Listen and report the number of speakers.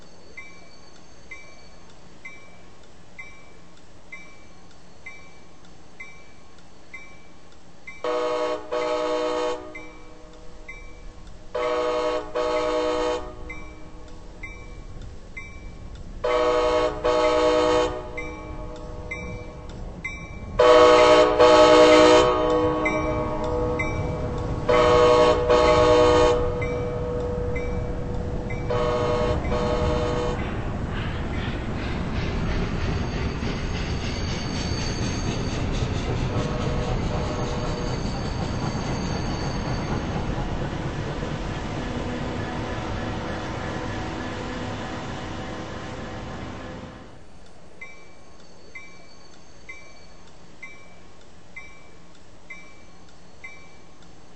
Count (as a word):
zero